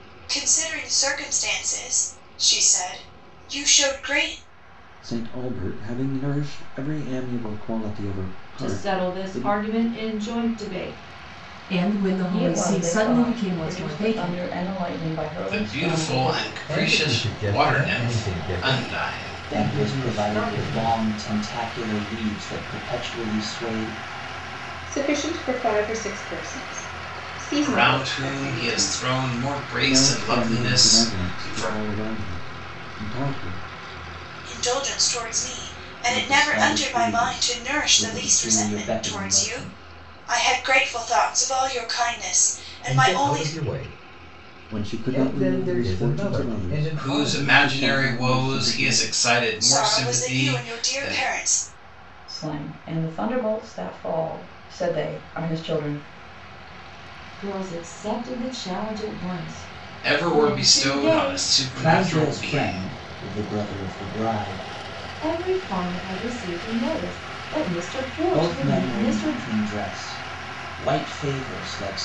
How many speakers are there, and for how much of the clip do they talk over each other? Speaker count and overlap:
9, about 38%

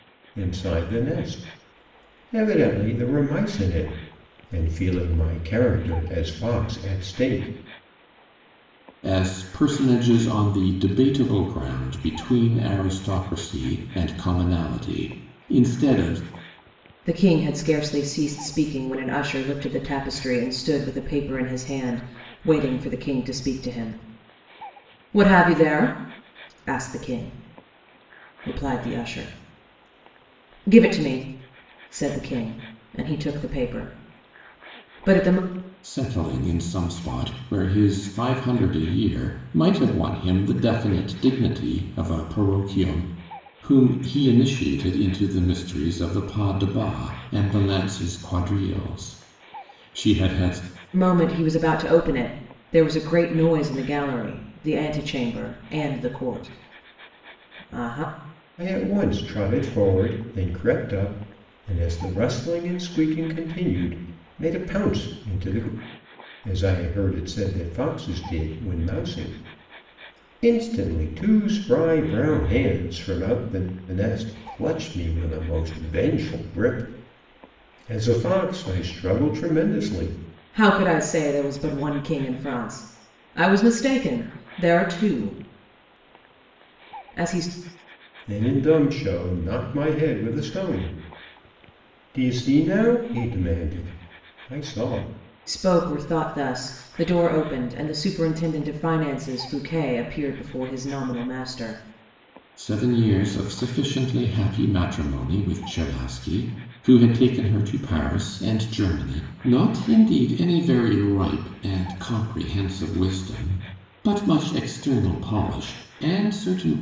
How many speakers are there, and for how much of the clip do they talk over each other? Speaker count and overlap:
3, no overlap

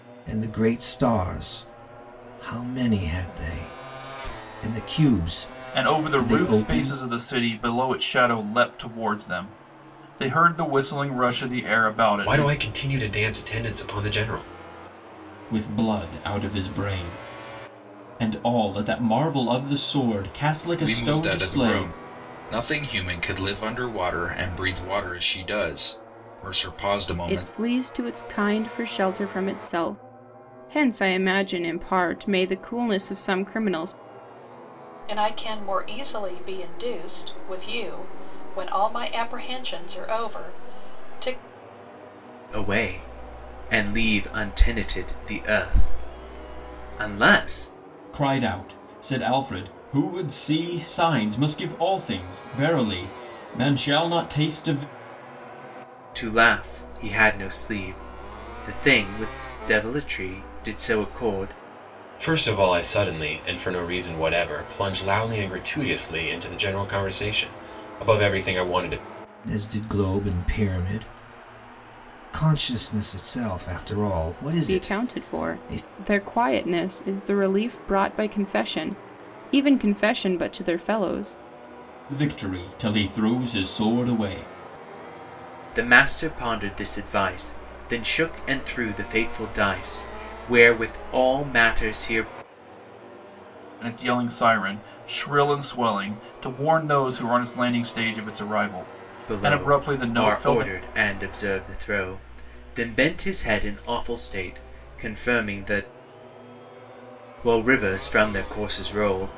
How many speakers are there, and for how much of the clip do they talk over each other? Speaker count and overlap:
8, about 5%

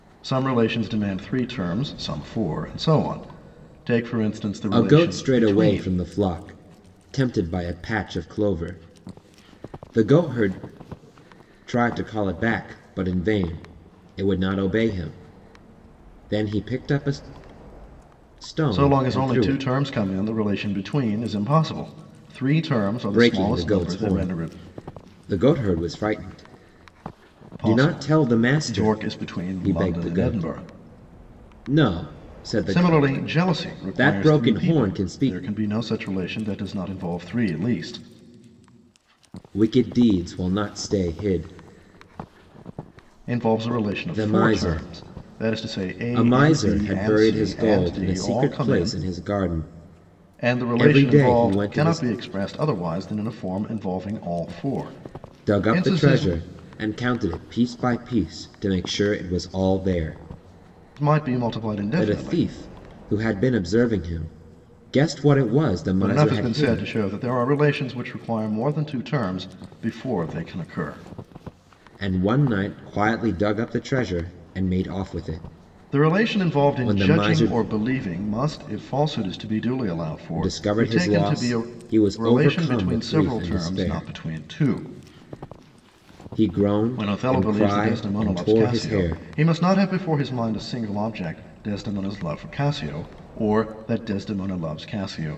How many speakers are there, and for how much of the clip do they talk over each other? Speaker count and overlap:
2, about 26%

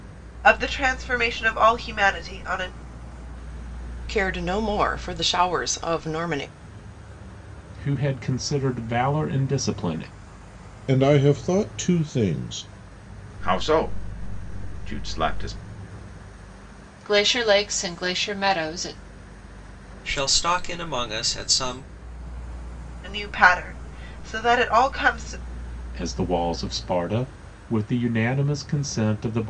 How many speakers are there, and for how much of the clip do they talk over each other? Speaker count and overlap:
7, no overlap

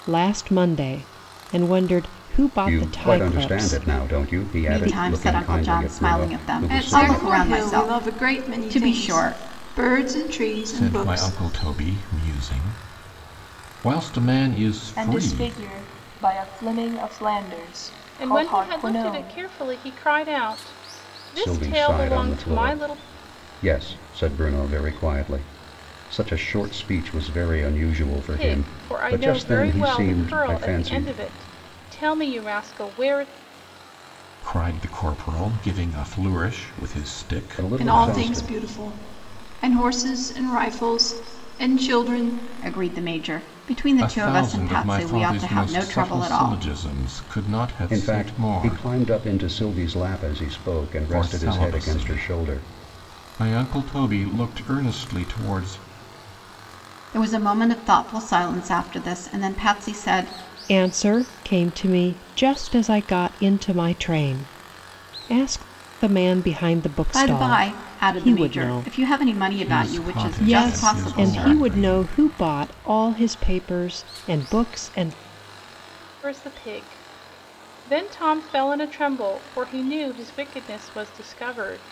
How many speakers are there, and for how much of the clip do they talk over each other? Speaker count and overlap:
7, about 30%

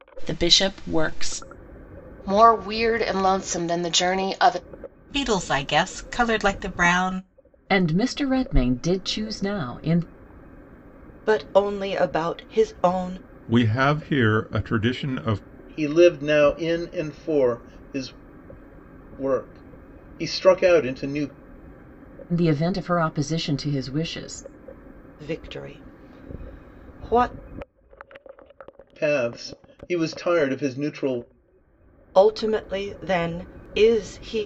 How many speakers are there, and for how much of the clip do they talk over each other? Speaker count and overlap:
7, no overlap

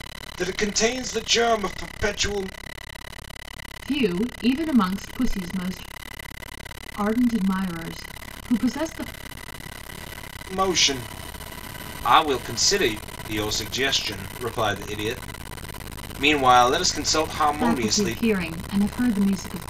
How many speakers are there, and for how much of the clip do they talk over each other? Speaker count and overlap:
2, about 4%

